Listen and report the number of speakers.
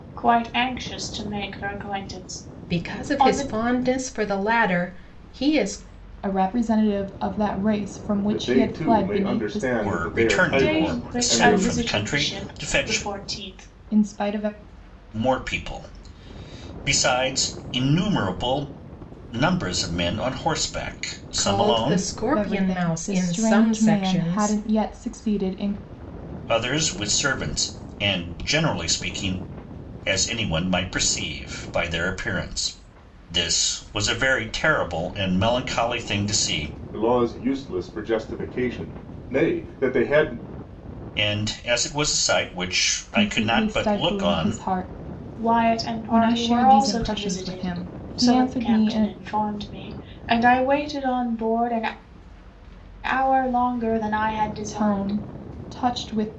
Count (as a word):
five